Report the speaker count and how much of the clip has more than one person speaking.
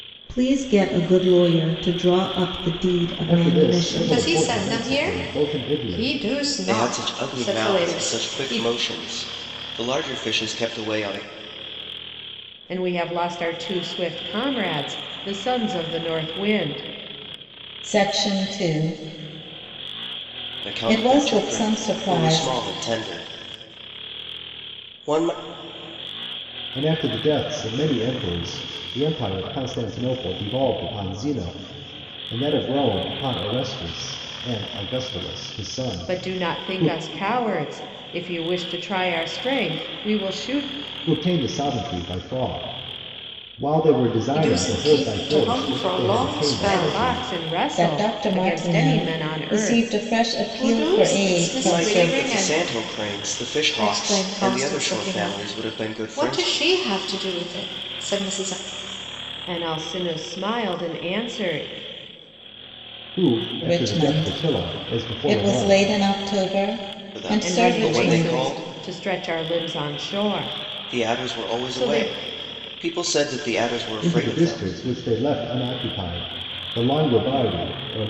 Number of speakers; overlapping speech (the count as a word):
five, about 31%